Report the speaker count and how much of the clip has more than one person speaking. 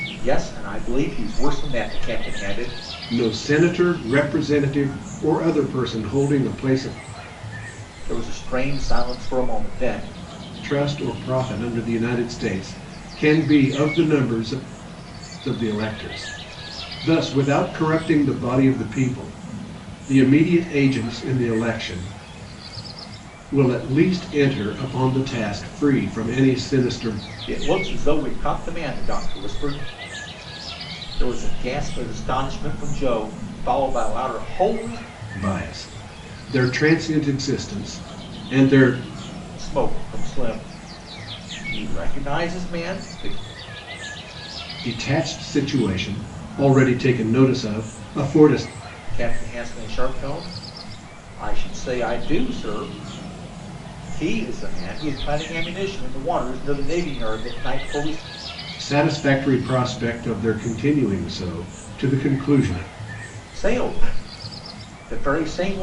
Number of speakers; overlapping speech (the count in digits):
2, no overlap